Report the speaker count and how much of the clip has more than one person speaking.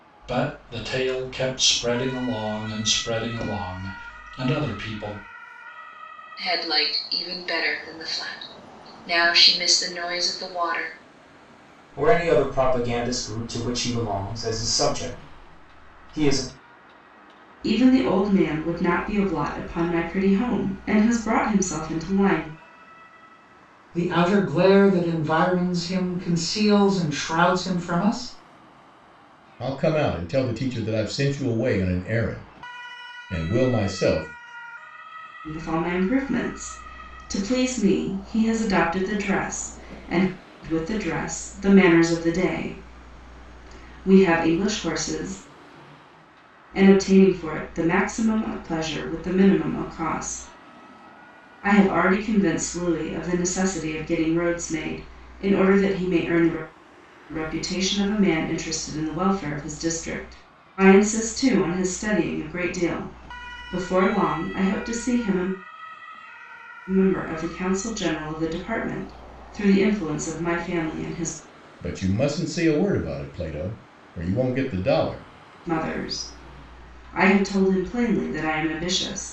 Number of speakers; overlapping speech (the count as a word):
six, no overlap